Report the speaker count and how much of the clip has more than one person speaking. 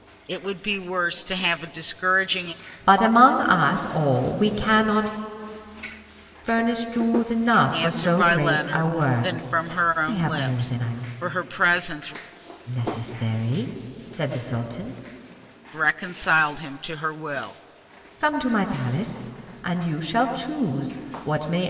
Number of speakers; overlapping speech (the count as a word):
two, about 16%